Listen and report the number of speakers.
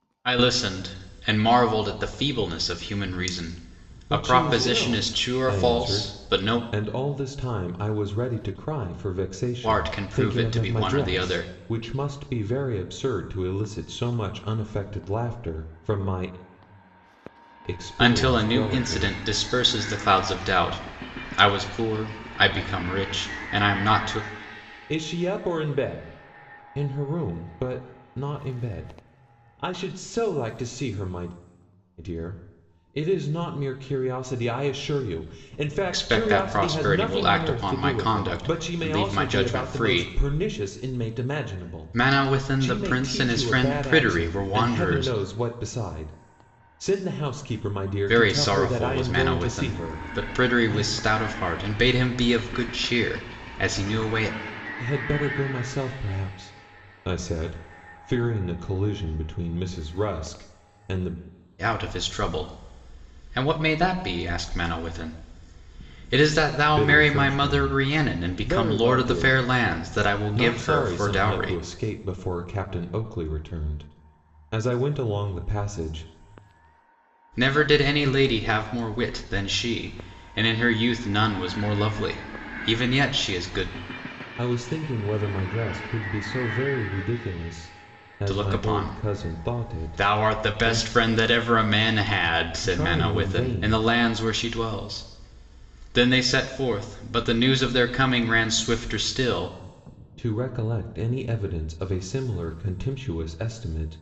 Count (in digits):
2